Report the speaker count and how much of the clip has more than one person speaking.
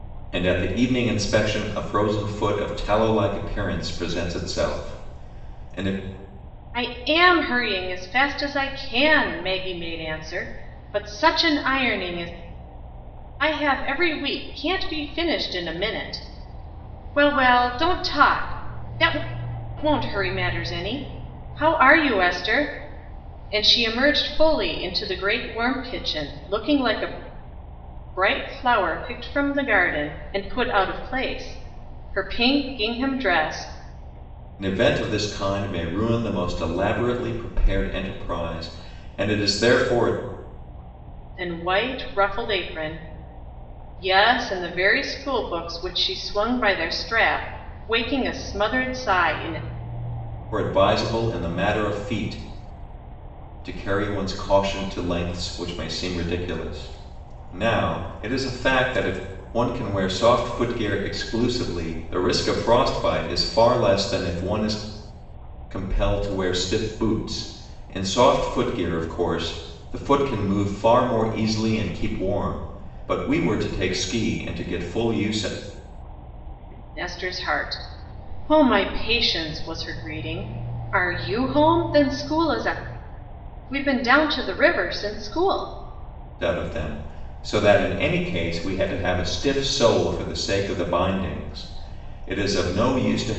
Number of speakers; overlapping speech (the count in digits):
2, no overlap